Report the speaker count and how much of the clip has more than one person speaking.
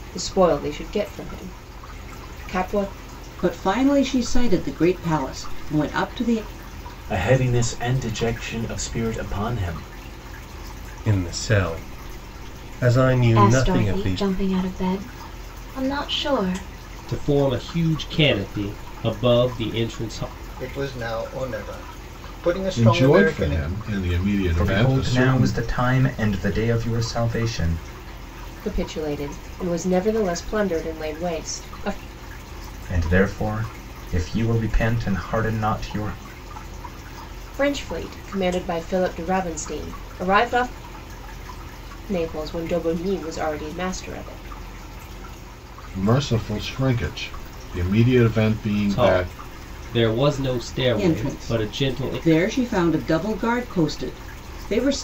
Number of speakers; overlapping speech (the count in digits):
9, about 8%